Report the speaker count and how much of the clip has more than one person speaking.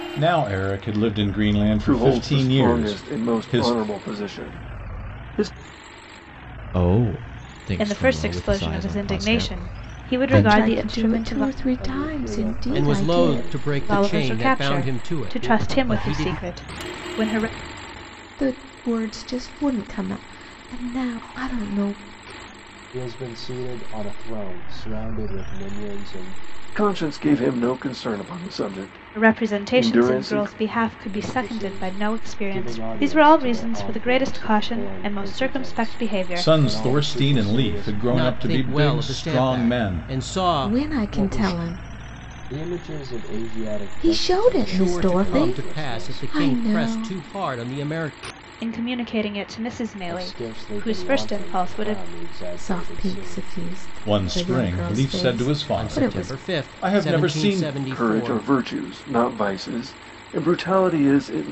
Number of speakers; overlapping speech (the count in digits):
7, about 52%